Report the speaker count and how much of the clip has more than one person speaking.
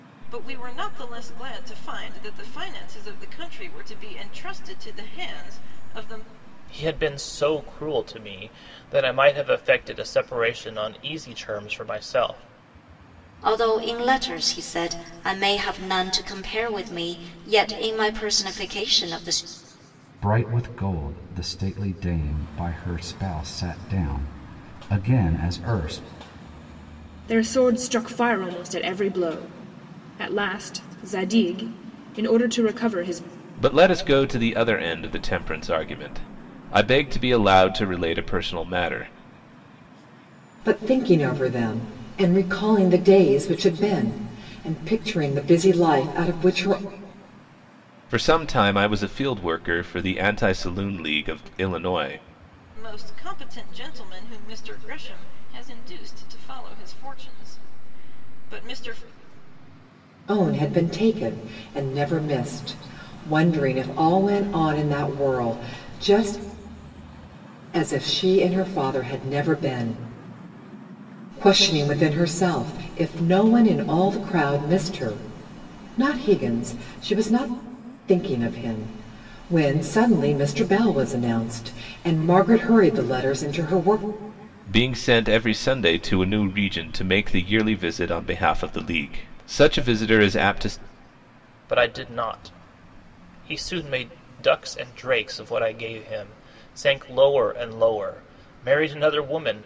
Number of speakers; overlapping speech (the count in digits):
7, no overlap